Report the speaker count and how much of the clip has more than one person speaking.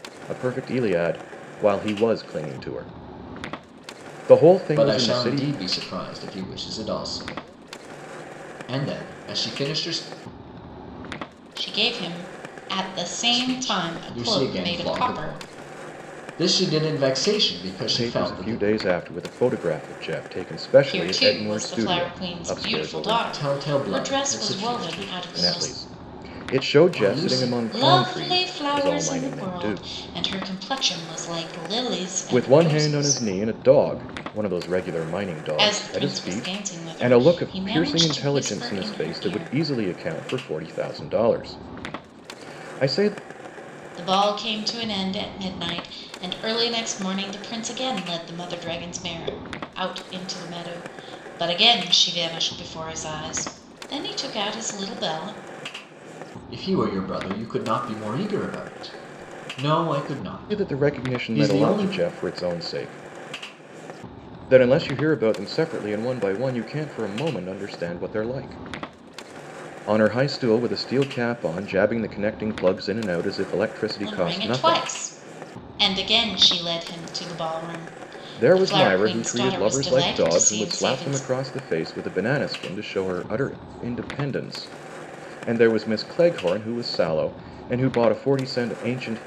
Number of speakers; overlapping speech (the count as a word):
three, about 25%